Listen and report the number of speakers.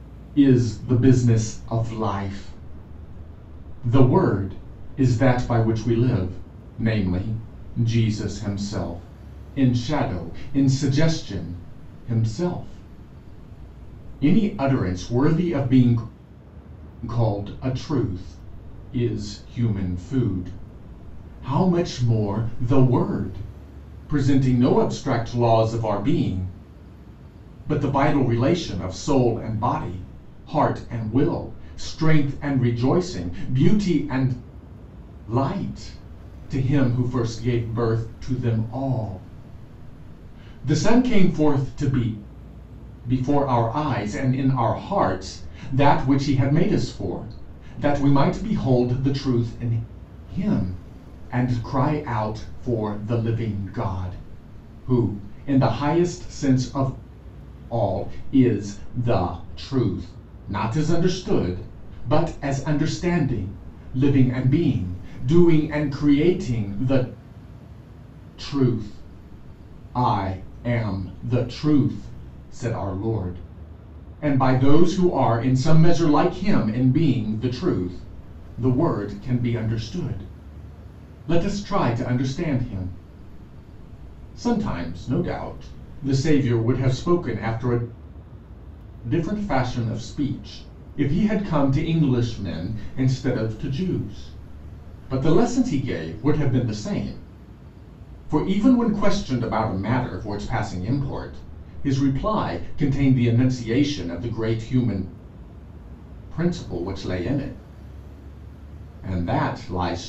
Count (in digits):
1